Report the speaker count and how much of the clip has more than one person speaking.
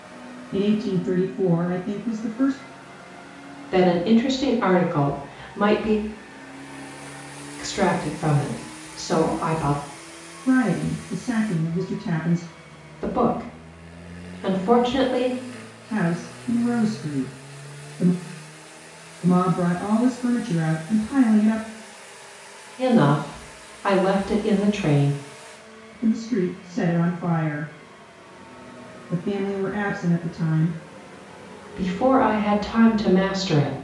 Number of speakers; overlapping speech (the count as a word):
two, no overlap